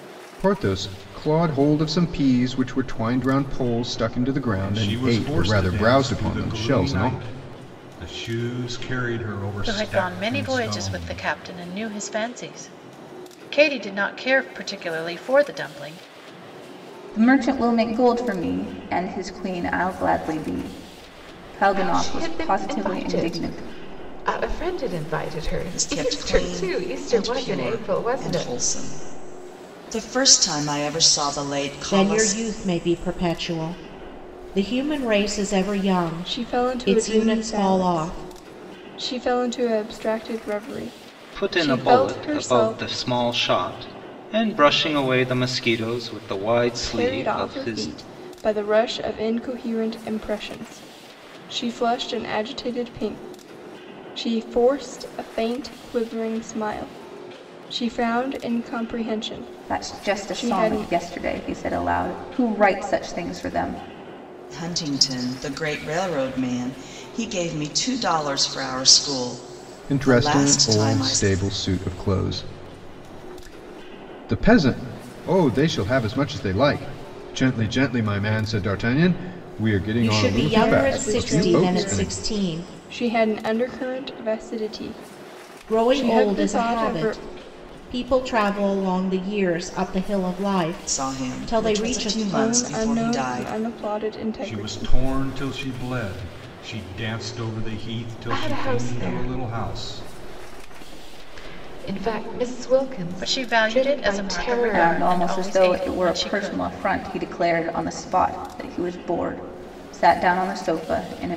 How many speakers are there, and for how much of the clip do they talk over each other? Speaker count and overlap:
nine, about 27%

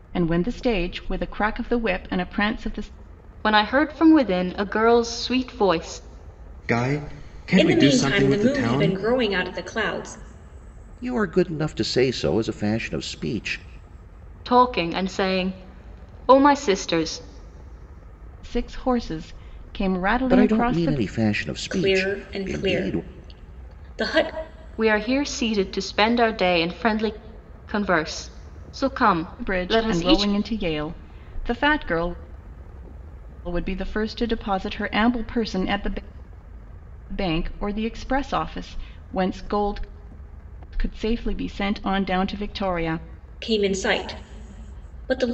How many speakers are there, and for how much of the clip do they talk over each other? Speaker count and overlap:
five, about 10%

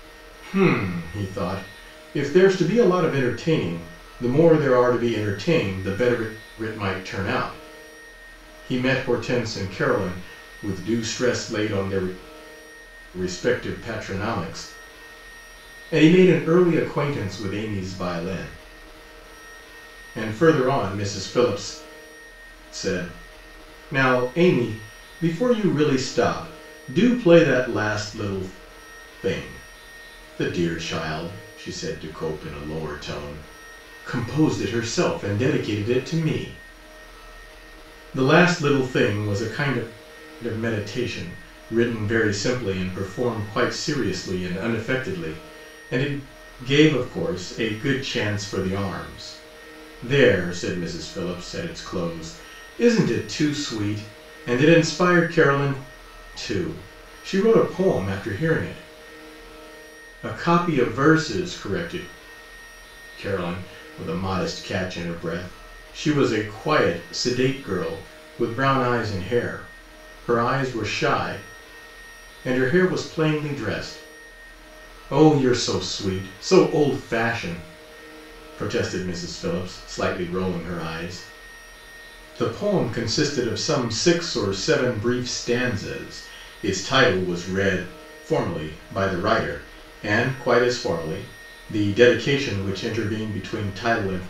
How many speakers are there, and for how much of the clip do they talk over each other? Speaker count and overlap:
one, no overlap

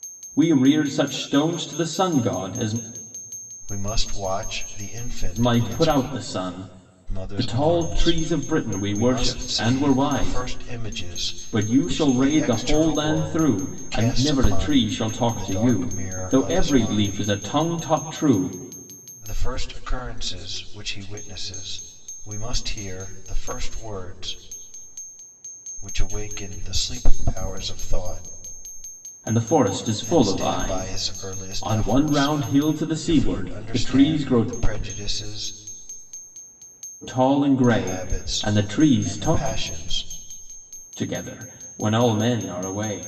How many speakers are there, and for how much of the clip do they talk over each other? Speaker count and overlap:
two, about 35%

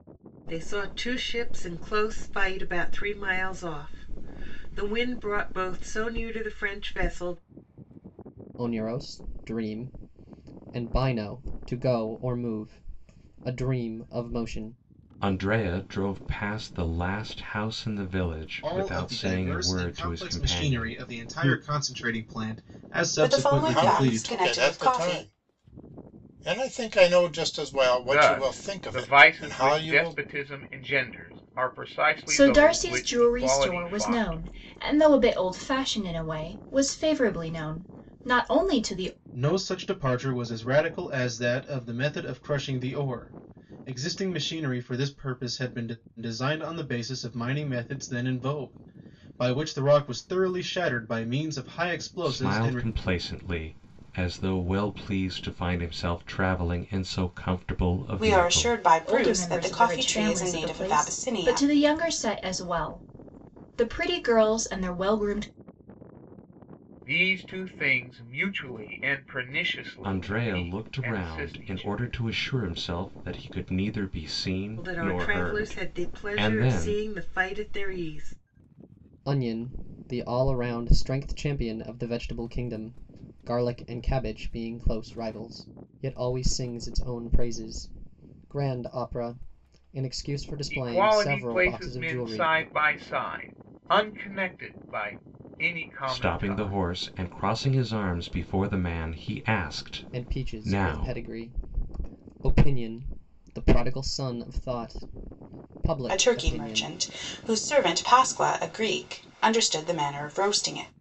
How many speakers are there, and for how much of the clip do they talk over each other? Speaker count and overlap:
eight, about 20%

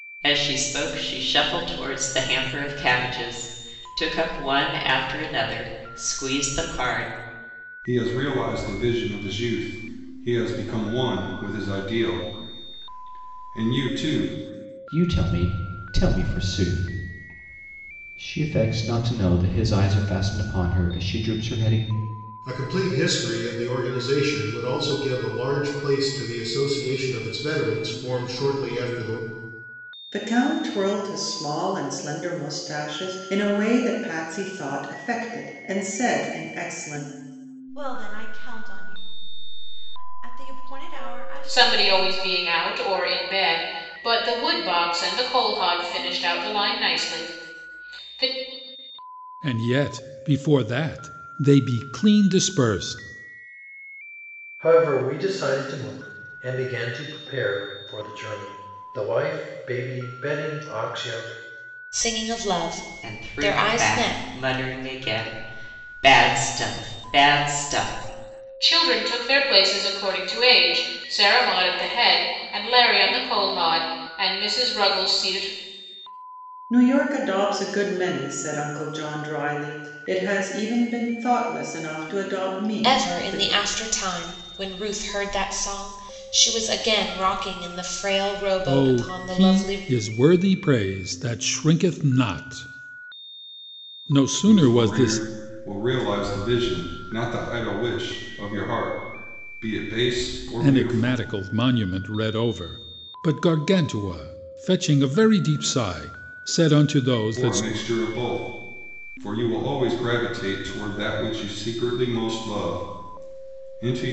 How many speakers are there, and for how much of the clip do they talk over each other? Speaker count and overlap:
ten, about 5%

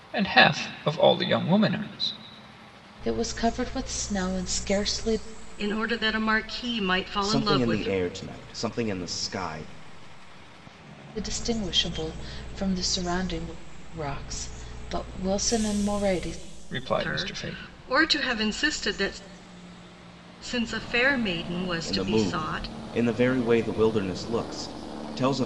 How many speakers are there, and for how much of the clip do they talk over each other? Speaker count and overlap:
four, about 10%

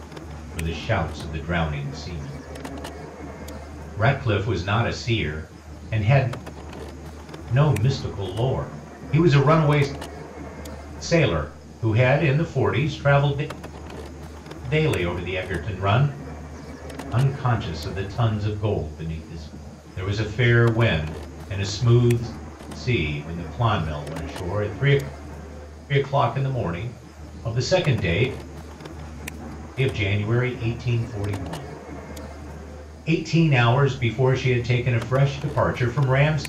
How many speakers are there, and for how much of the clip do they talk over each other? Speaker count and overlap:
one, no overlap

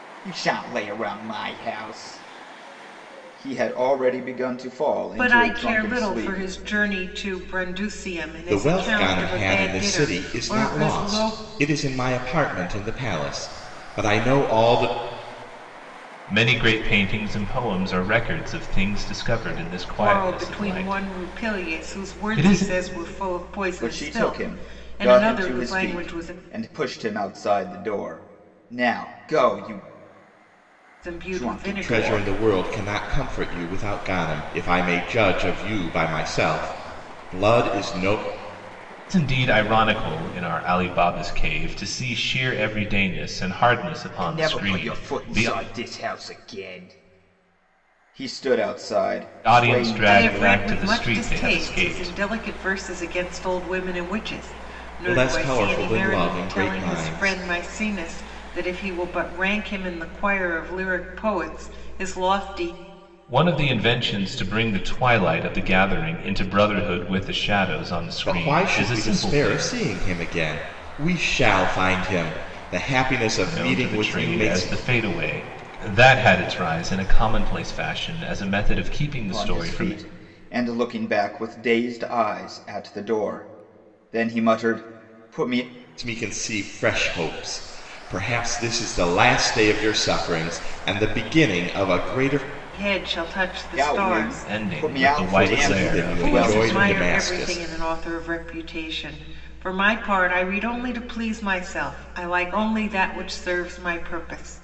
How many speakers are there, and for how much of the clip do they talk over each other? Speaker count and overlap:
four, about 24%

